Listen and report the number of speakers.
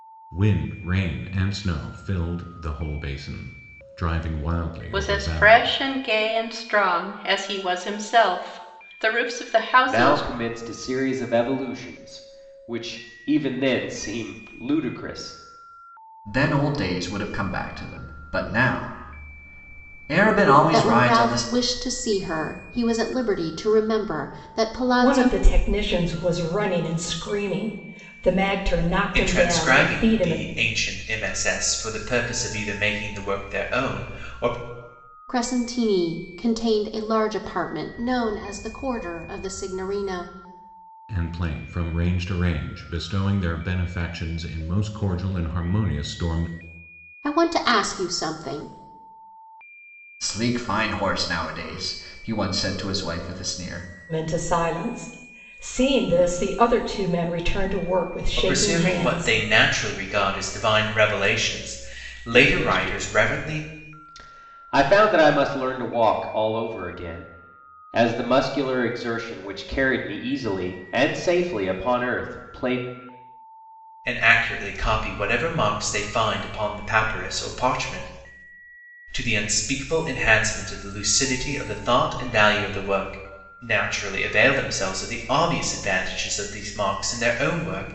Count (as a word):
seven